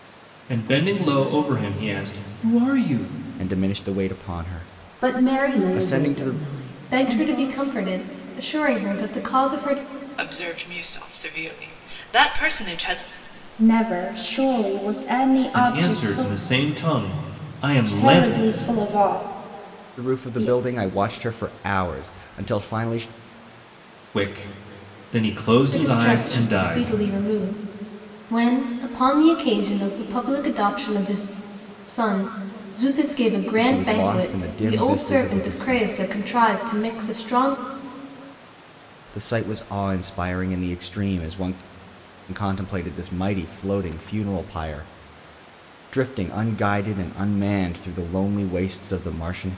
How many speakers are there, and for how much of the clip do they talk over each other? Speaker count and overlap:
6, about 16%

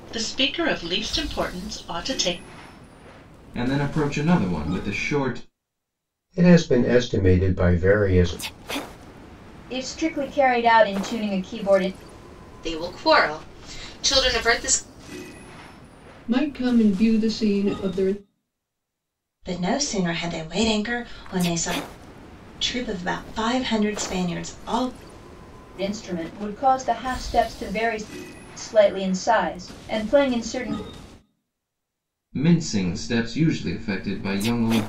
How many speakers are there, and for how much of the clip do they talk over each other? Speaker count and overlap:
7, no overlap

